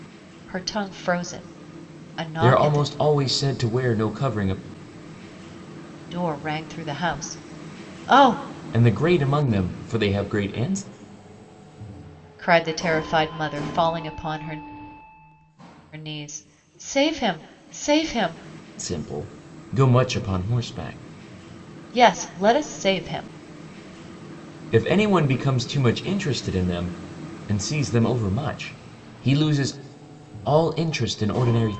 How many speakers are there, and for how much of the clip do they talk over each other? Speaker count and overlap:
2, about 2%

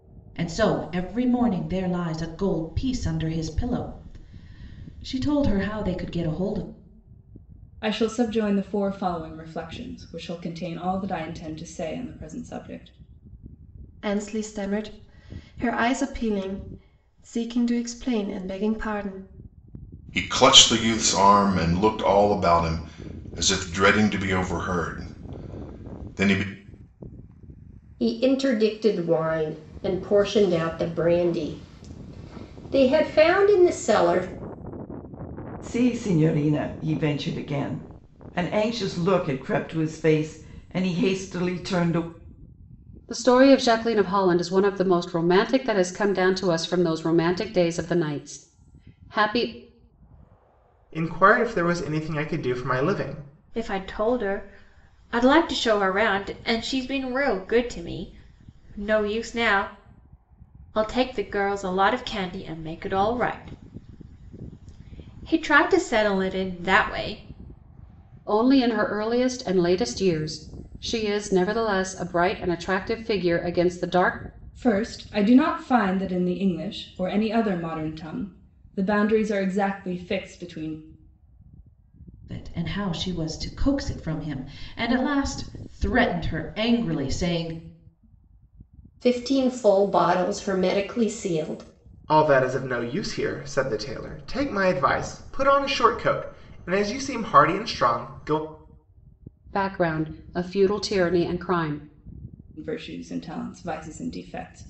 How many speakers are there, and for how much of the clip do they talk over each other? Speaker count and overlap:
9, no overlap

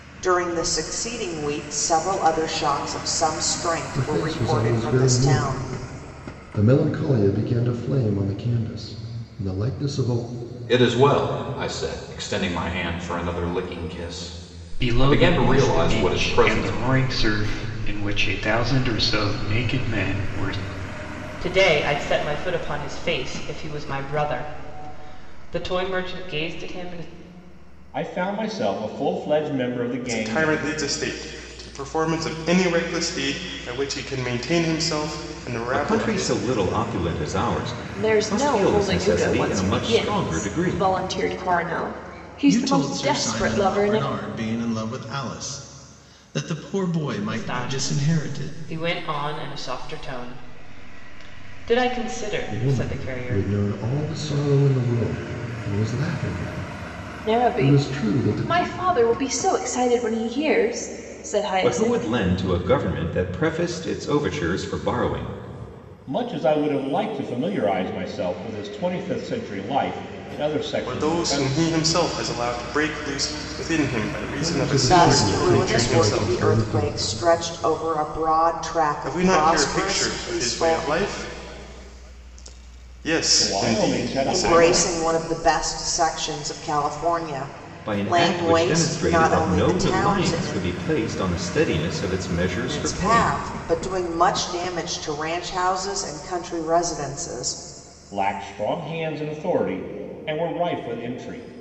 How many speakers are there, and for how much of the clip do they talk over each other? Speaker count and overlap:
10, about 25%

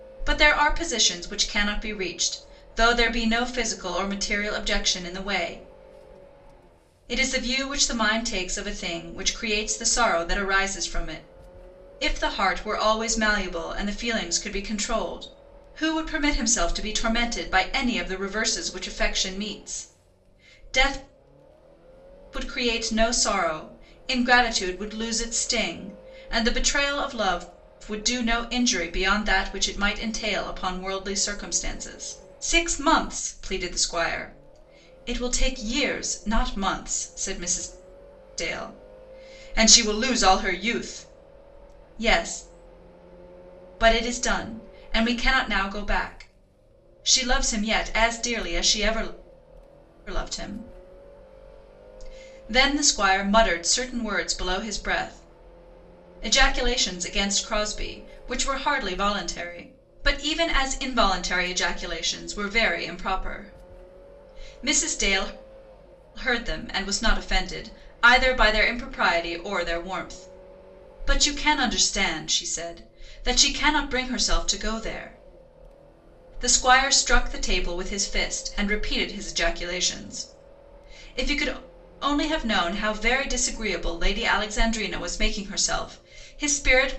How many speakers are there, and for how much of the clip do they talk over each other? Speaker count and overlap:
1, no overlap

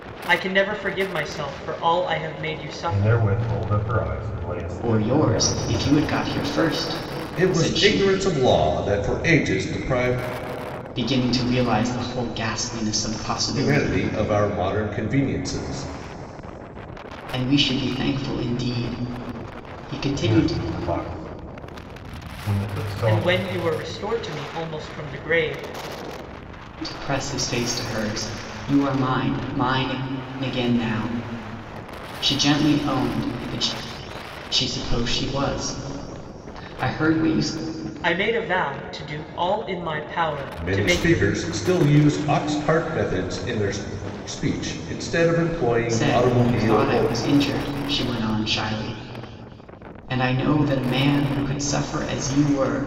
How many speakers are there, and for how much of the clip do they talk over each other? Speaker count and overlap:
4, about 11%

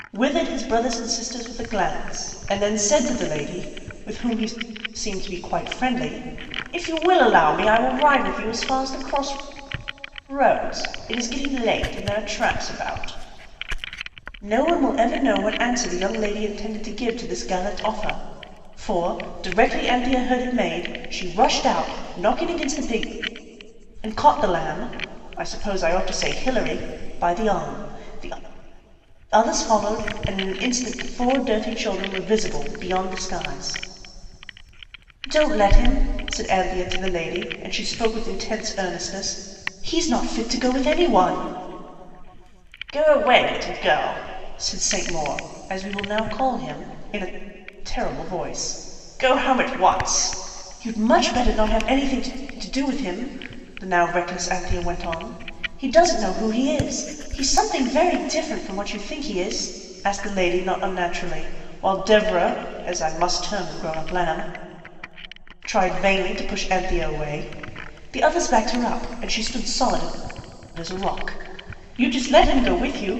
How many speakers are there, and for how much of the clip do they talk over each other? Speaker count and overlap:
1, no overlap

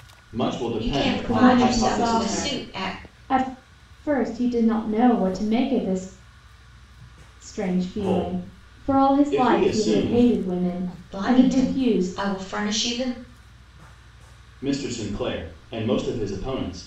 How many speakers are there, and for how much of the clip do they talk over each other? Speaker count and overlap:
3, about 34%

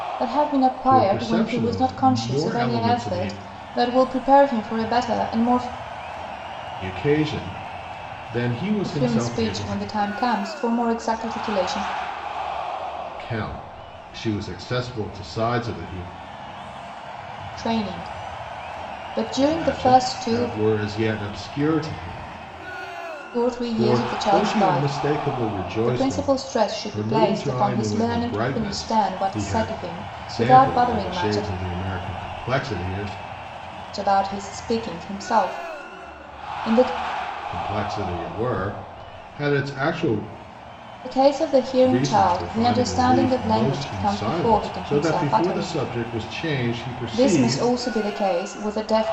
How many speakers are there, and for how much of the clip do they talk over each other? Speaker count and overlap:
2, about 31%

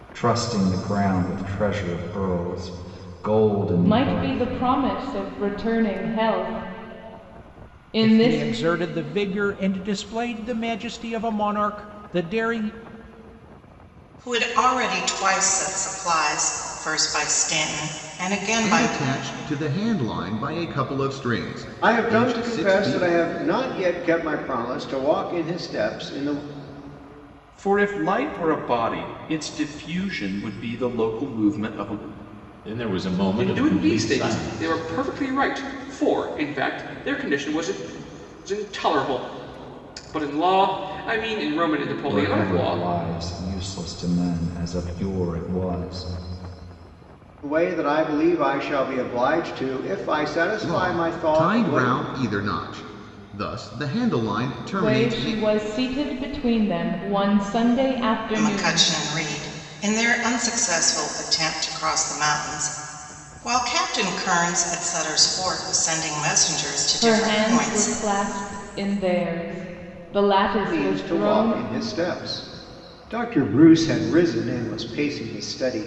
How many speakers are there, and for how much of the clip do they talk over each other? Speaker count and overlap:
9, about 13%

